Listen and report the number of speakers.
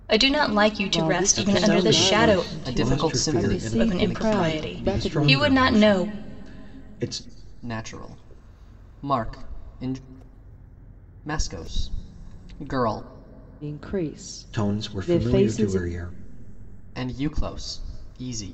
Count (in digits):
4